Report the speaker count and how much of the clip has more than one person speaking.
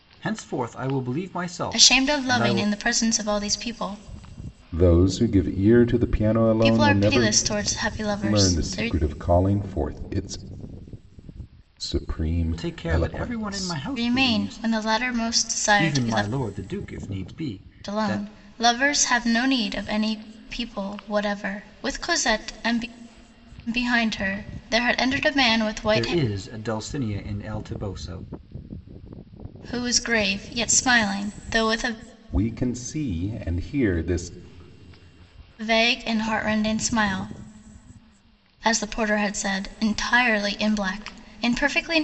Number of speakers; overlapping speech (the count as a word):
three, about 14%